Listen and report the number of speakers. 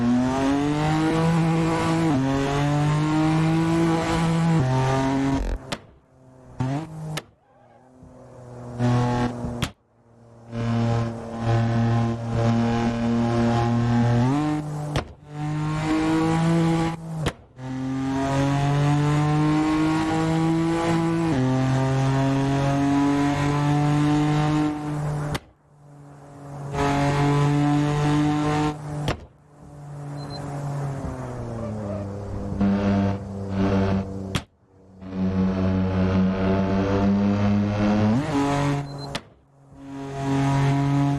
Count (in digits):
0